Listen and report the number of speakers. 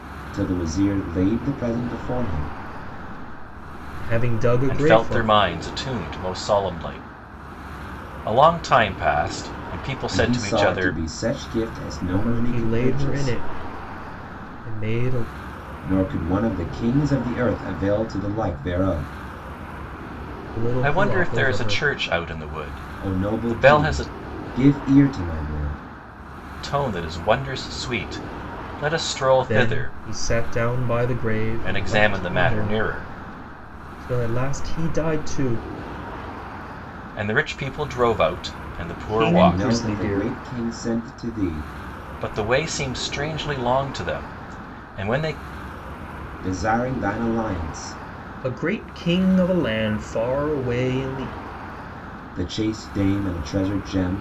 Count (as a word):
three